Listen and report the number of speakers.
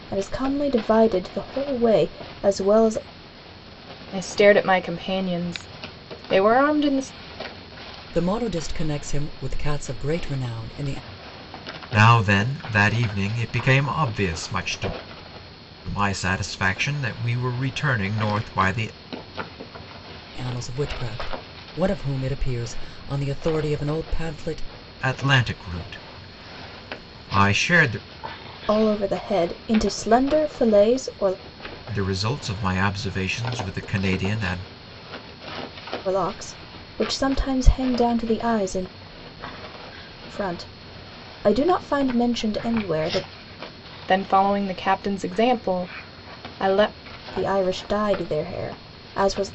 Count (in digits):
4